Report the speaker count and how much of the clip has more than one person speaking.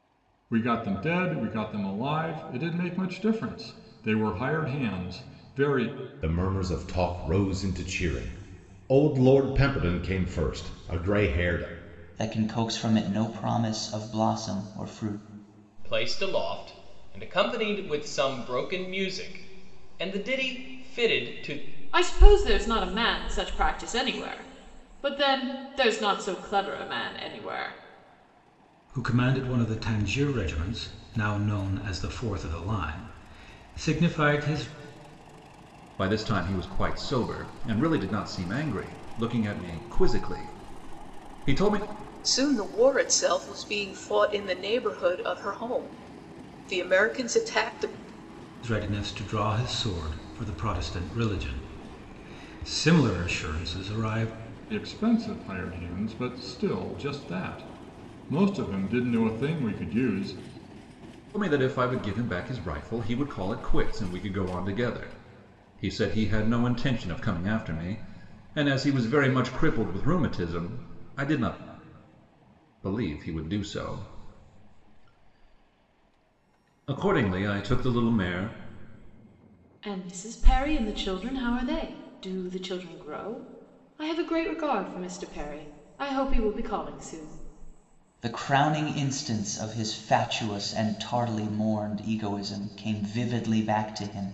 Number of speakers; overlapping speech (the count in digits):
8, no overlap